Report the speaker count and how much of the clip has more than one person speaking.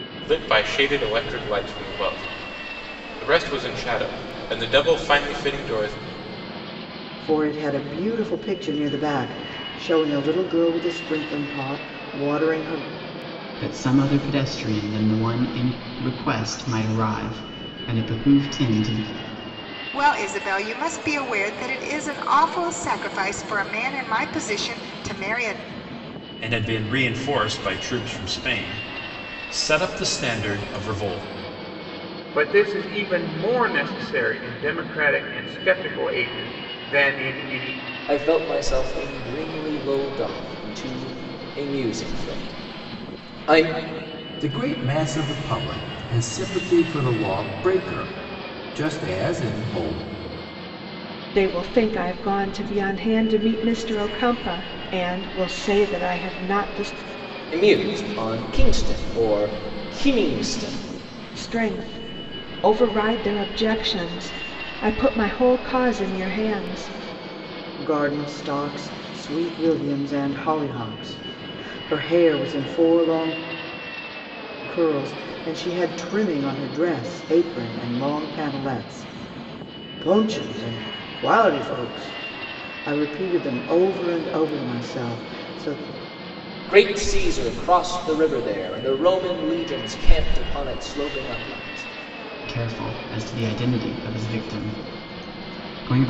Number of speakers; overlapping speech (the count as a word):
nine, no overlap